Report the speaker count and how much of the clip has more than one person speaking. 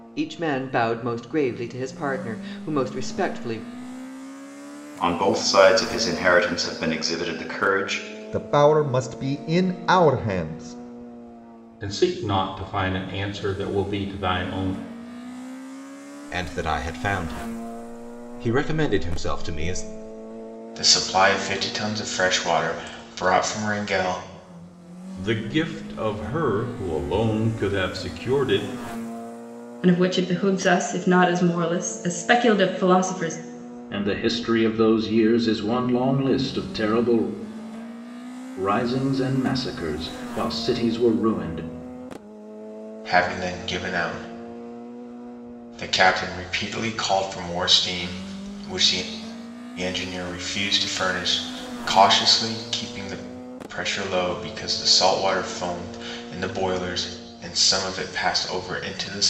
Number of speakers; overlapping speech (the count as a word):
nine, no overlap